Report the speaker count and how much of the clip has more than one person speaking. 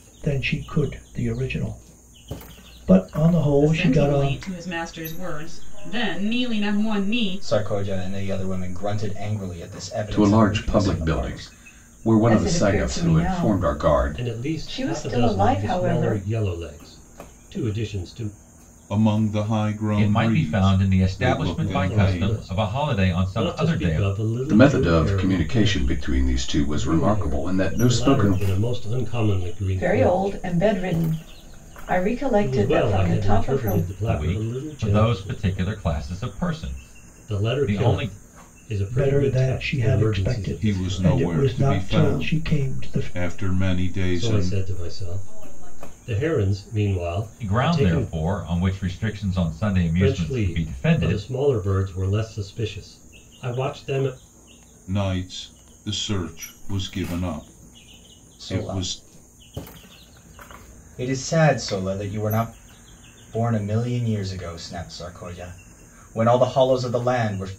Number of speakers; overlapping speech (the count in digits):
9, about 50%